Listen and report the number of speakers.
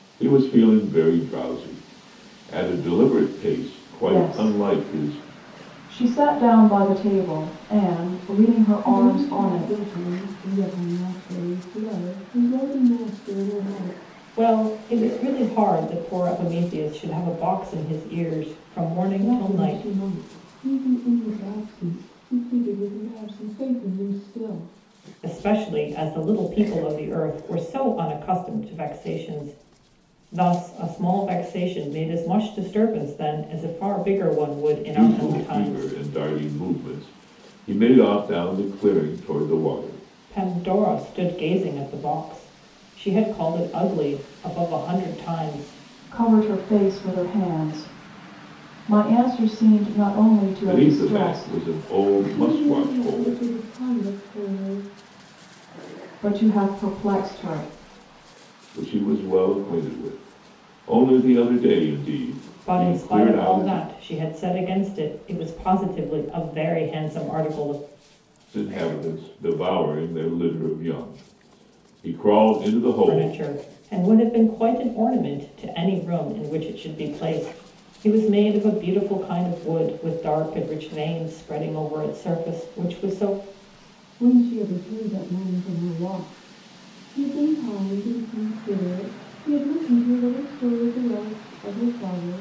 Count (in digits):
4